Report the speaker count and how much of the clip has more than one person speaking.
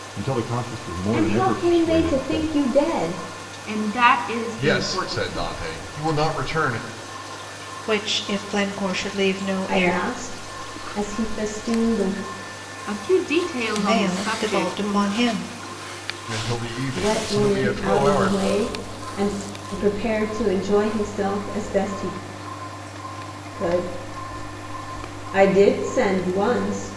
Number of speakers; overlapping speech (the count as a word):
five, about 21%